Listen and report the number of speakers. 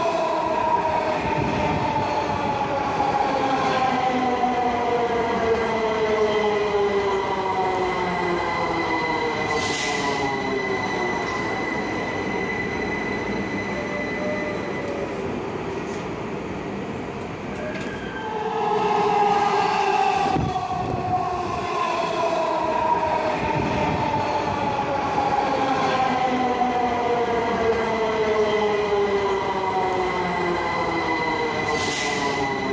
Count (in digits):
0